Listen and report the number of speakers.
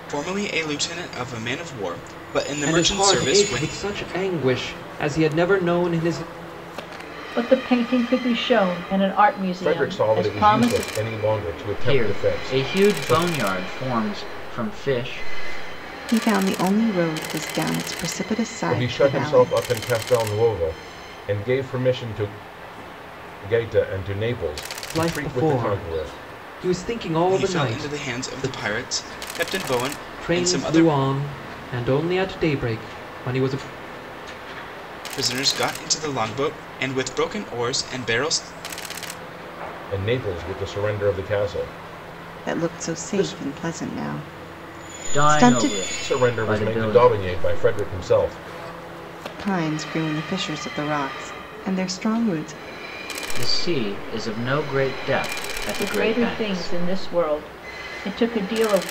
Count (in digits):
6